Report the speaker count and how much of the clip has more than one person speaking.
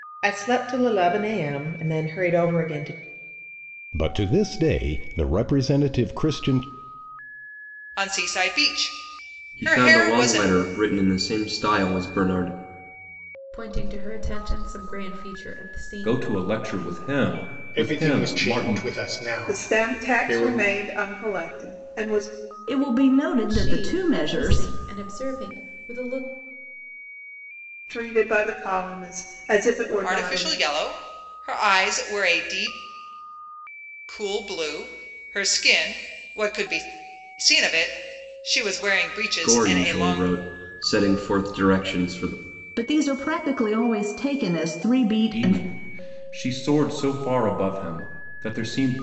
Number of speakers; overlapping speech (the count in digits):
9, about 14%